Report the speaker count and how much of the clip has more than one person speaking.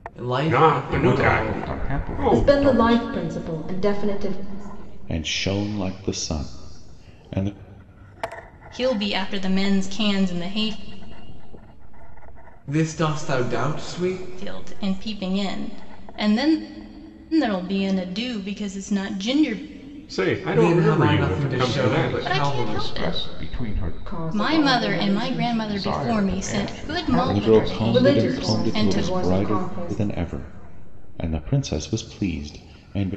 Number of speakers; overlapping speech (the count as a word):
eight, about 55%